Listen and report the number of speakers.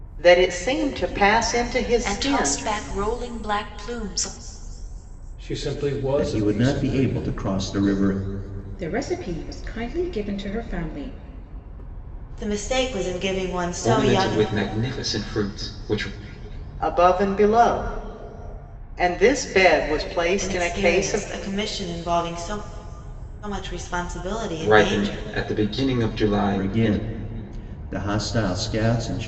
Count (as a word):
seven